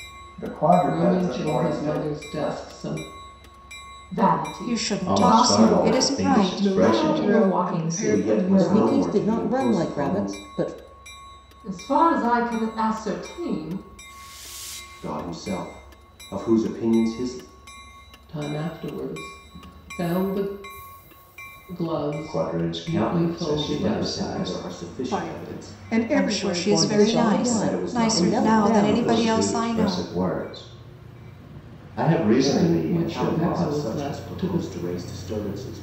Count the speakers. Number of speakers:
9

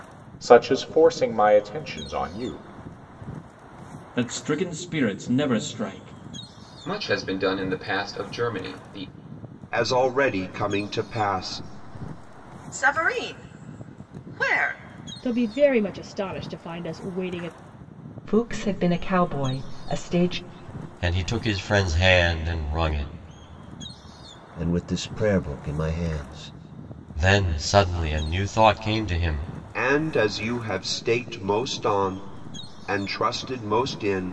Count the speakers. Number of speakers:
9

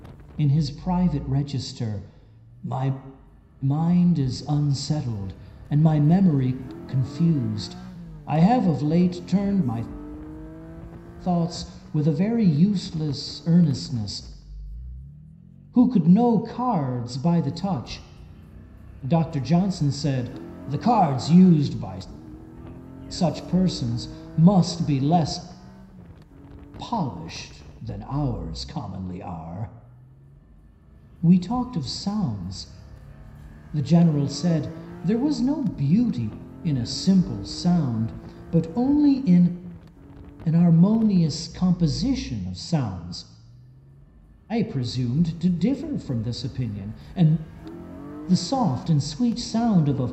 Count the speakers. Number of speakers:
1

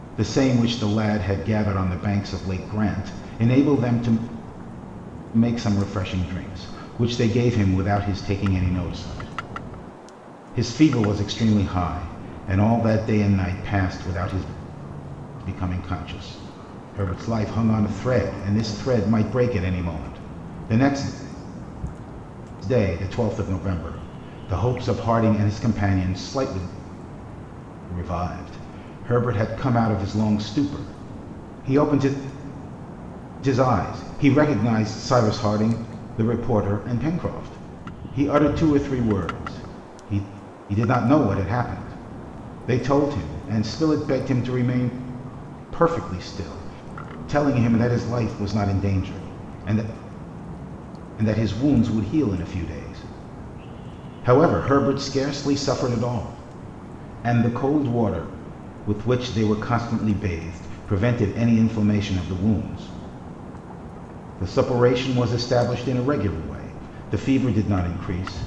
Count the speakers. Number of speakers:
1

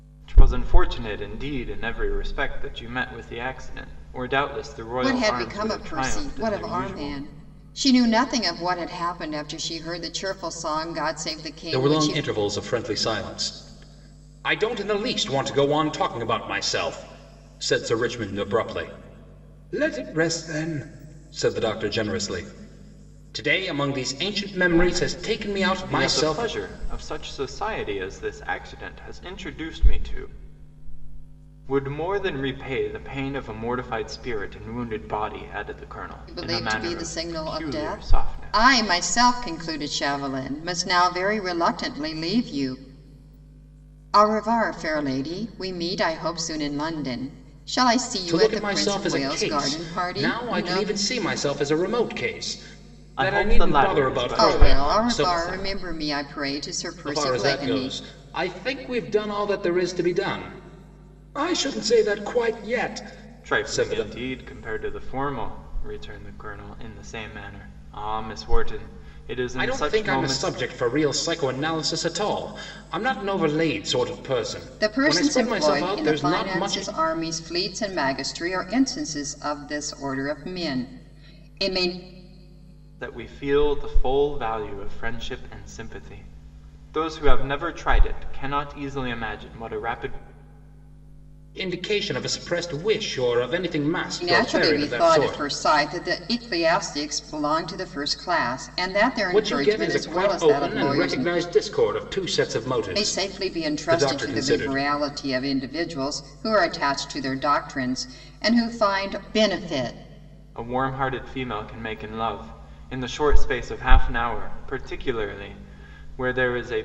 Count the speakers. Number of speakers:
3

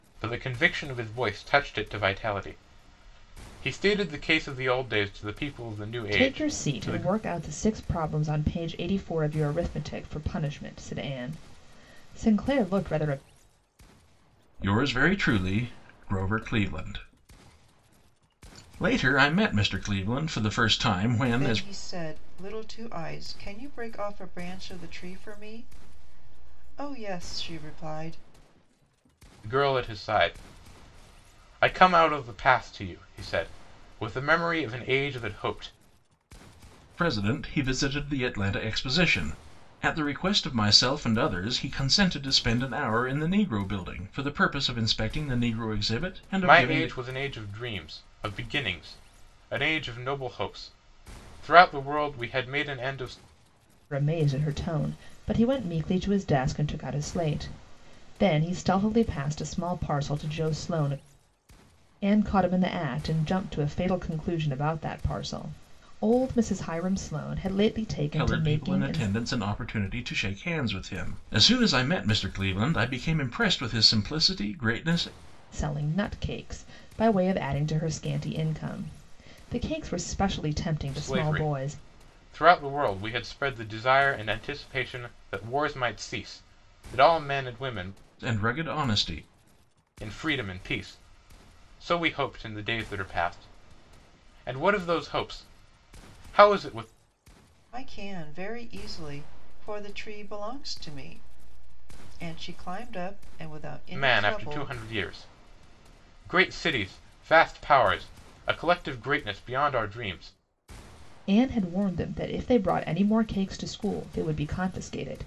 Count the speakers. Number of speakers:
4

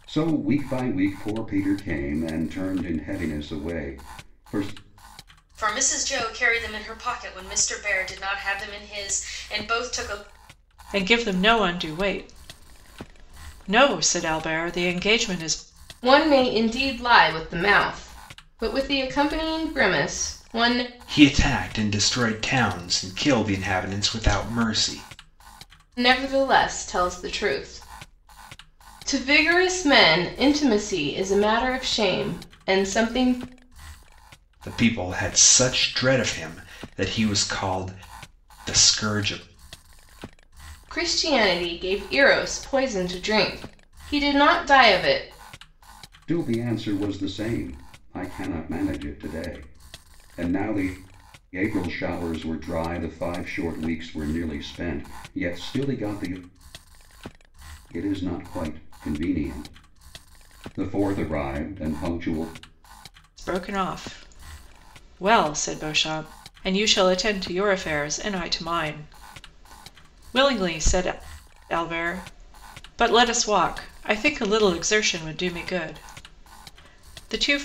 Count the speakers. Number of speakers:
5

